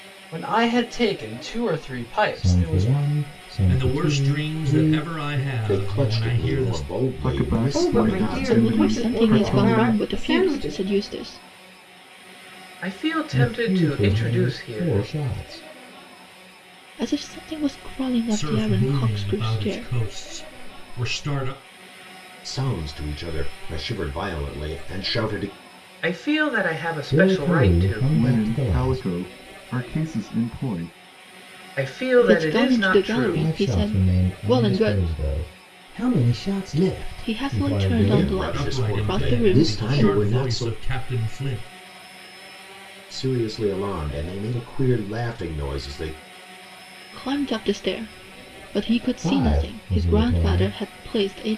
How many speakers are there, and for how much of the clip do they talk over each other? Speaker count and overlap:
8, about 40%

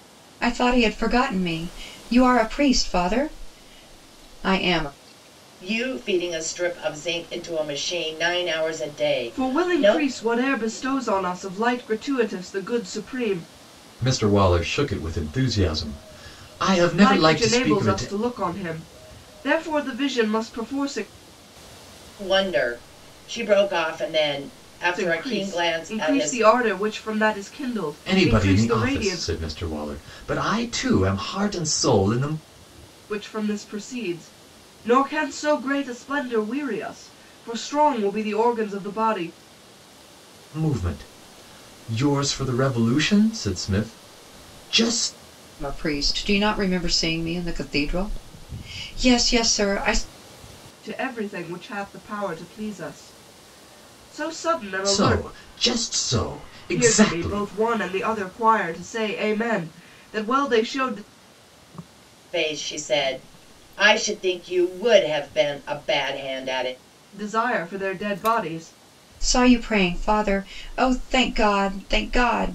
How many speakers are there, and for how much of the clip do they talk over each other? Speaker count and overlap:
4, about 8%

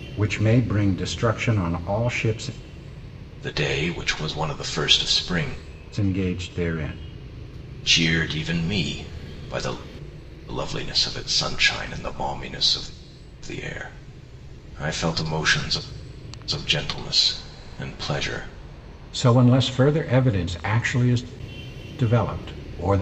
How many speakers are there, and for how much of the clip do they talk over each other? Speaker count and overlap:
2, no overlap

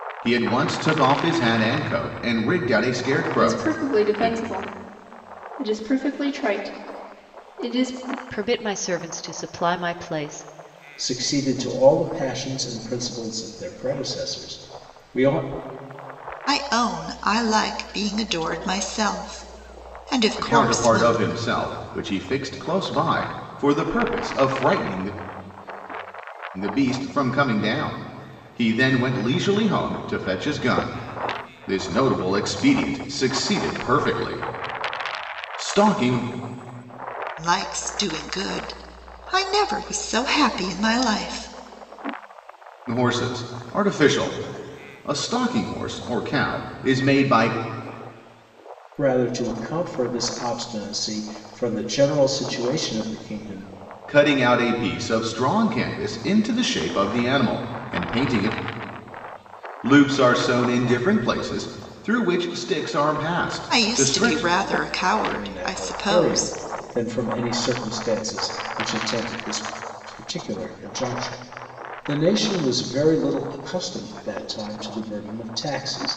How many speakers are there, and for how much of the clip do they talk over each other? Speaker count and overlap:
5, about 5%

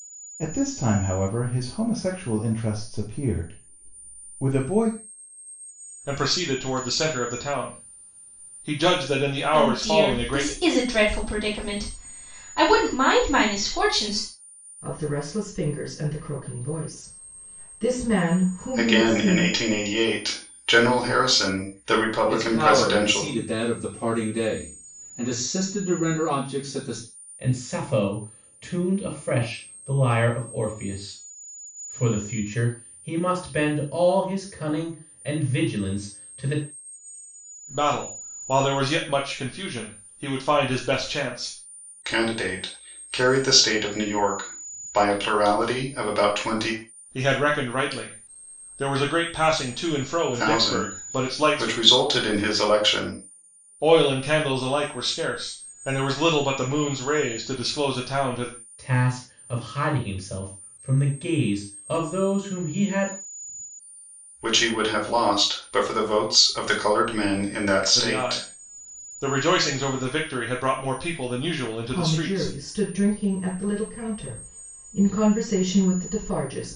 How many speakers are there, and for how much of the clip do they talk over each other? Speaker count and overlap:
7, about 7%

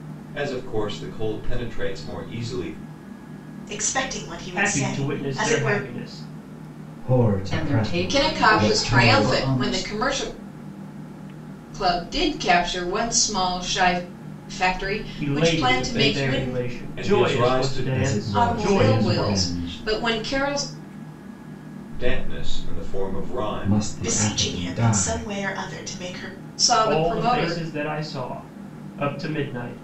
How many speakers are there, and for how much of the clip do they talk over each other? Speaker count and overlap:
6, about 37%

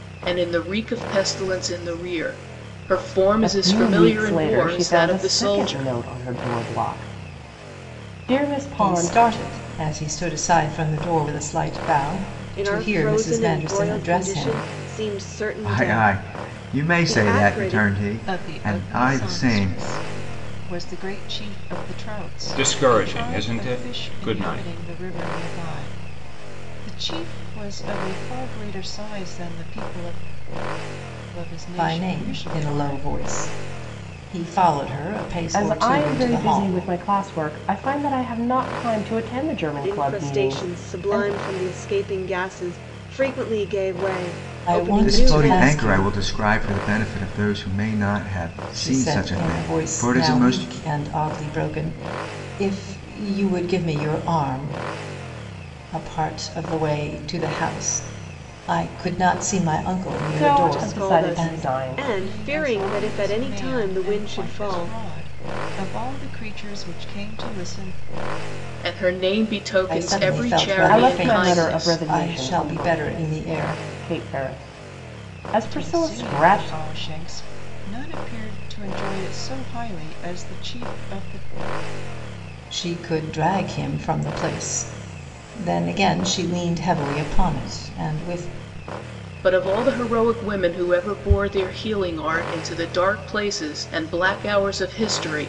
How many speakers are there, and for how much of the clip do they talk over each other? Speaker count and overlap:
7, about 30%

